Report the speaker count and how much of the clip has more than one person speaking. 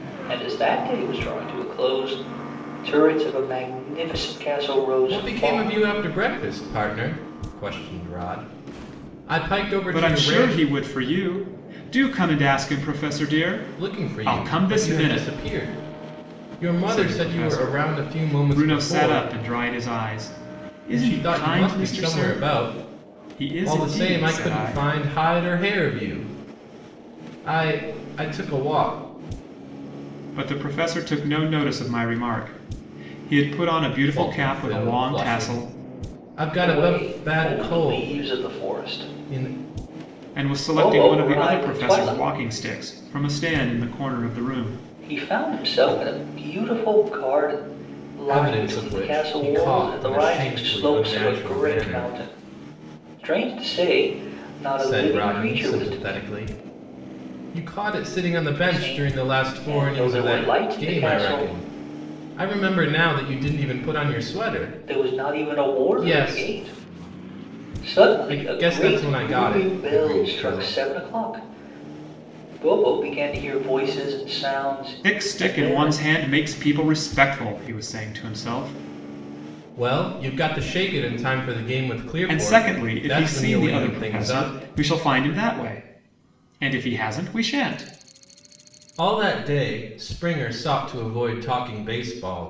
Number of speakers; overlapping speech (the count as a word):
three, about 34%